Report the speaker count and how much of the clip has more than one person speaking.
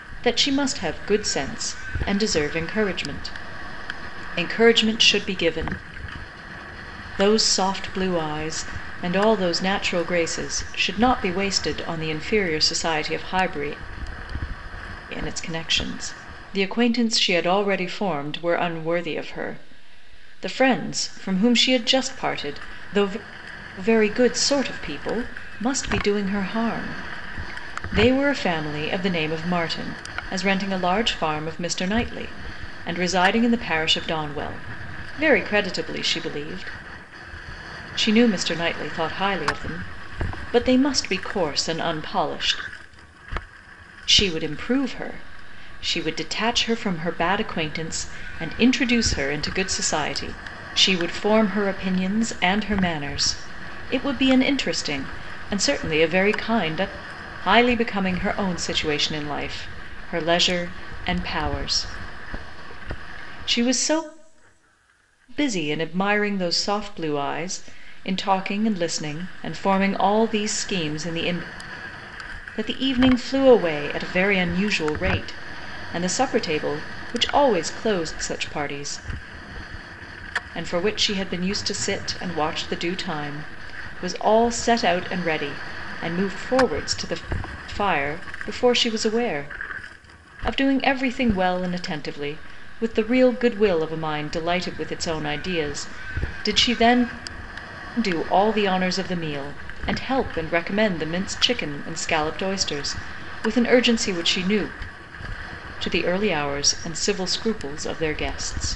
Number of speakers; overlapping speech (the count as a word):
one, no overlap